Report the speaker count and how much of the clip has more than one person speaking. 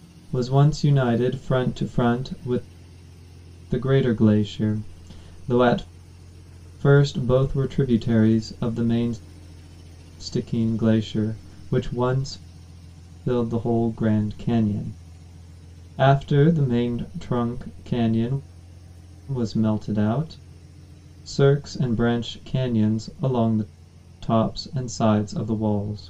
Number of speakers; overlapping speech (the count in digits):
1, no overlap